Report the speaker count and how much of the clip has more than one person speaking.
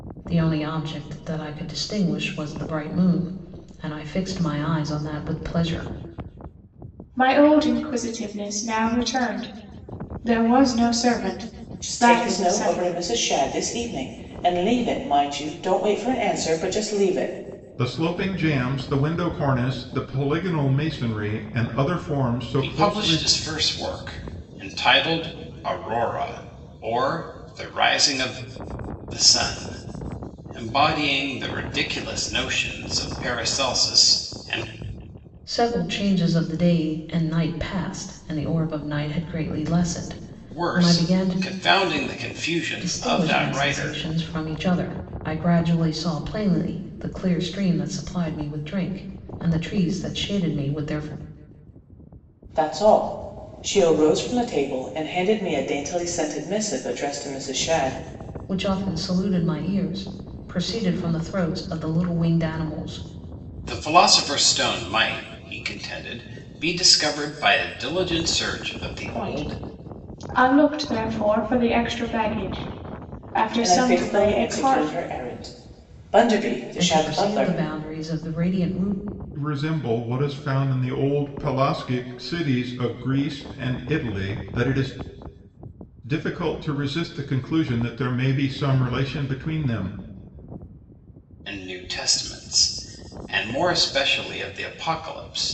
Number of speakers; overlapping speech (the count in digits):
5, about 7%